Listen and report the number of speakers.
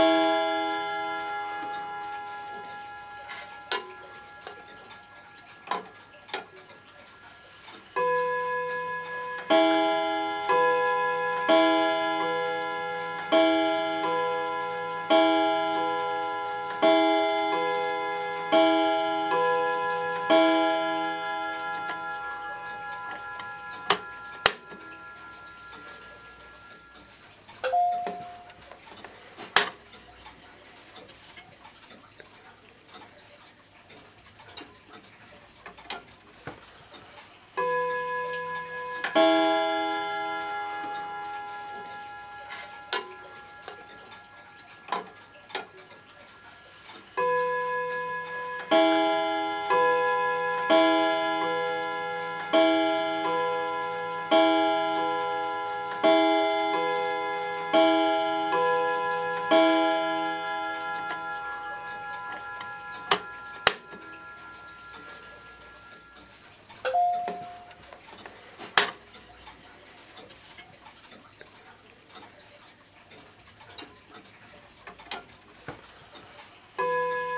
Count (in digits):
0